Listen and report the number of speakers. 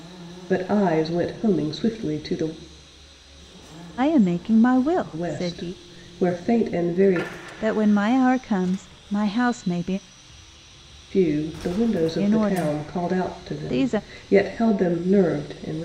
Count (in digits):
2